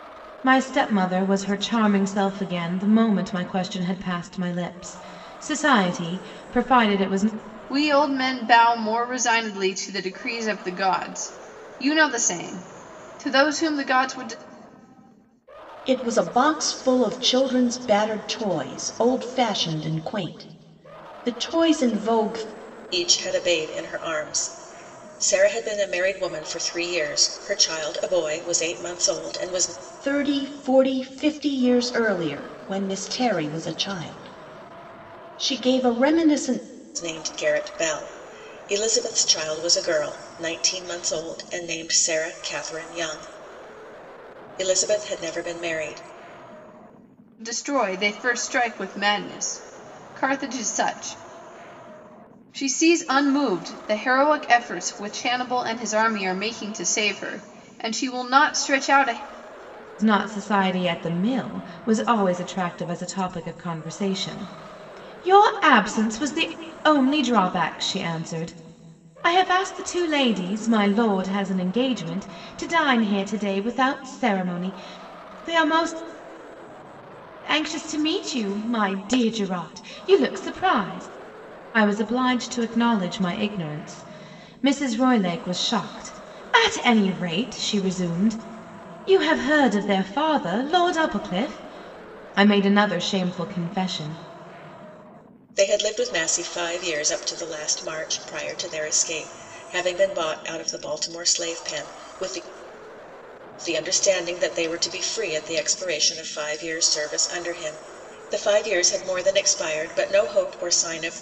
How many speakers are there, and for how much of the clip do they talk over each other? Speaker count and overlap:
4, no overlap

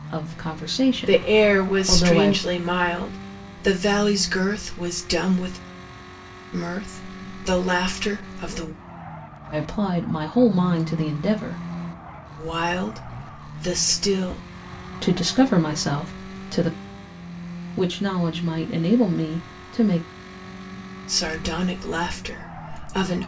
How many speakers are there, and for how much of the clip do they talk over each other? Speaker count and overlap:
2, about 6%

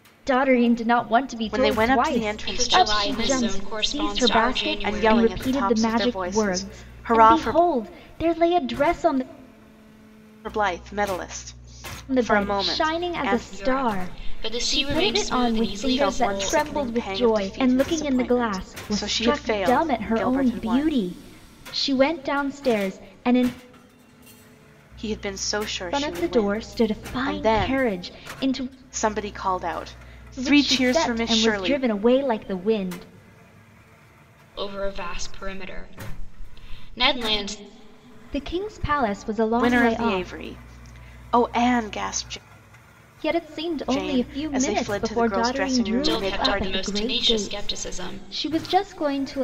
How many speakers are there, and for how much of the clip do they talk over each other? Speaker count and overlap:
3, about 47%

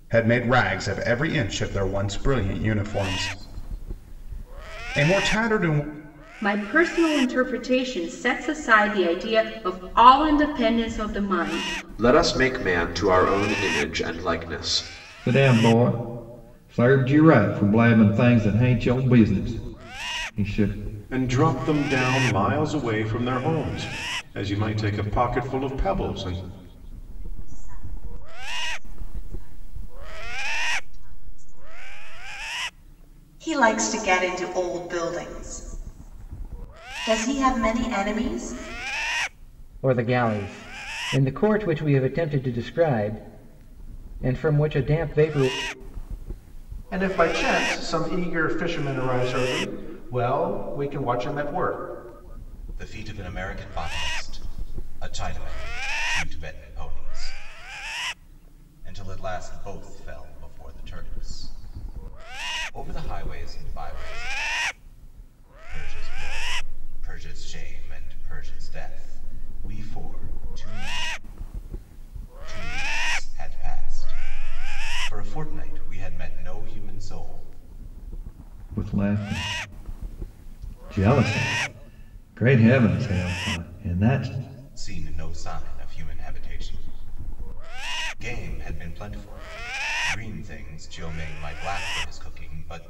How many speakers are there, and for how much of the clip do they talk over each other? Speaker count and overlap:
10, no overlap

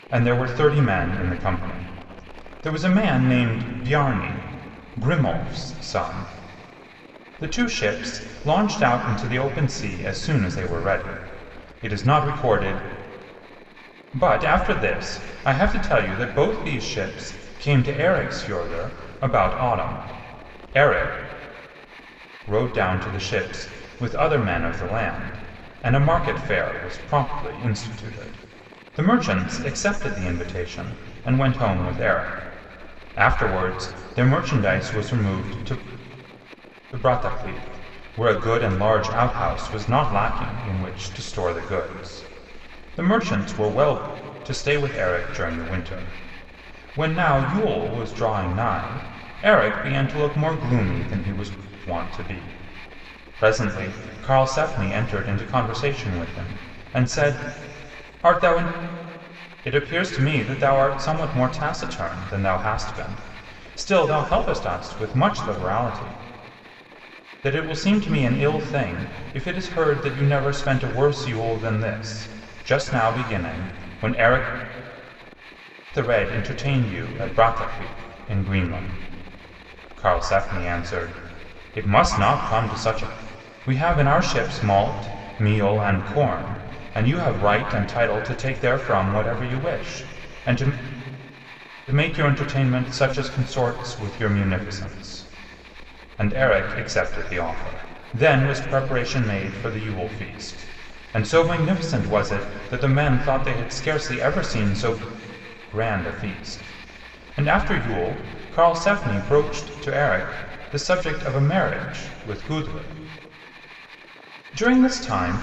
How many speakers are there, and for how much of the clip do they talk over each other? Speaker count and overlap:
1, no overlap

